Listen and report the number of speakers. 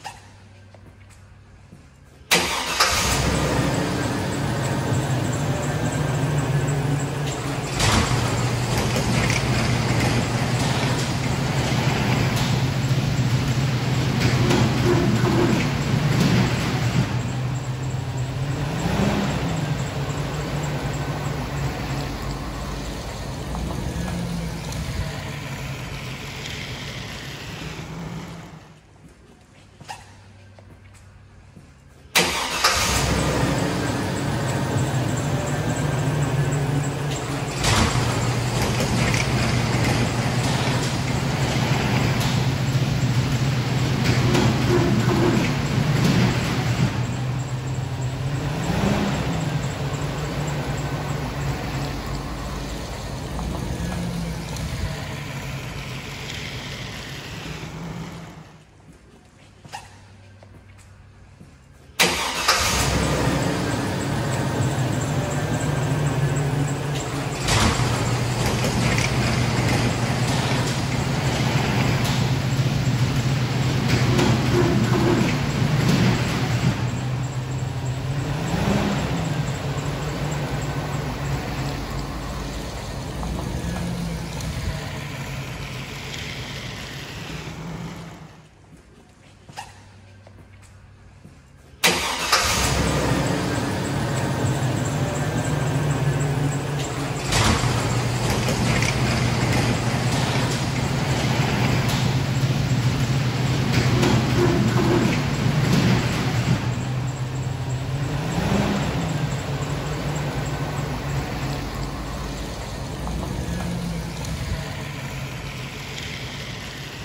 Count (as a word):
zero